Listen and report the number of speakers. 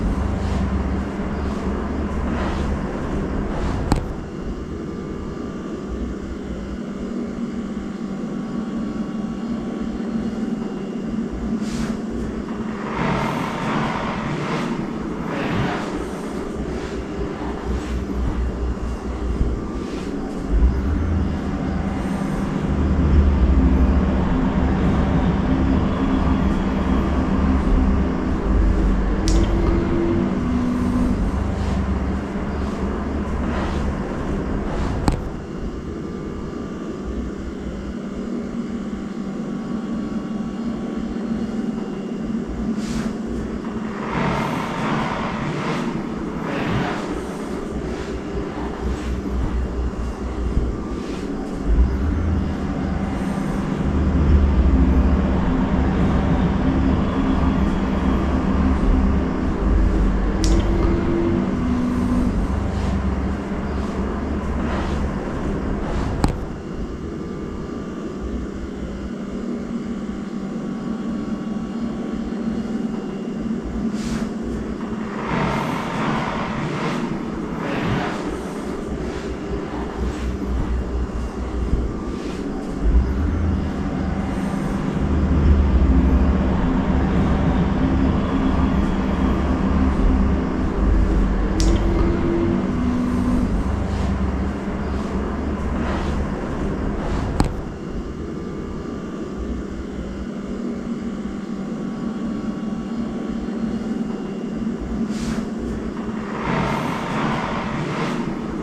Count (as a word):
zero